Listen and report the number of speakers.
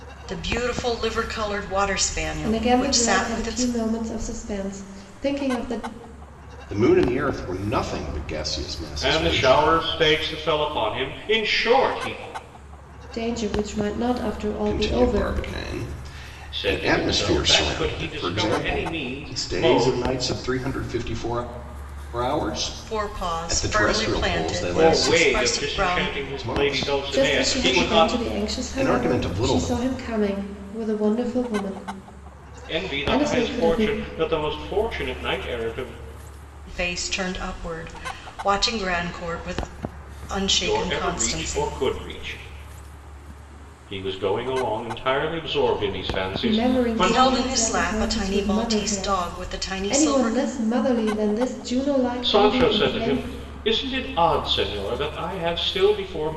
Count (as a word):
four